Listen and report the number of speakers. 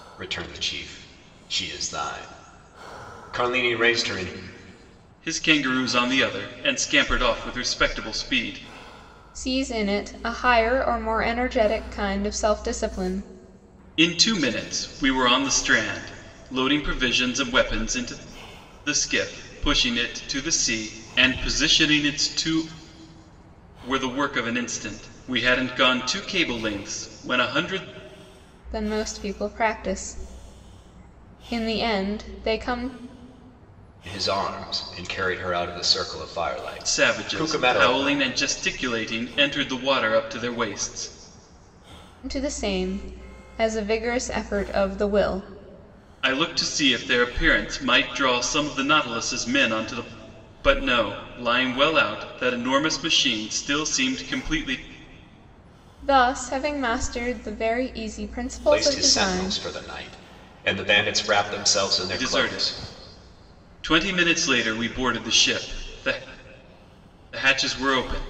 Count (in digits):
3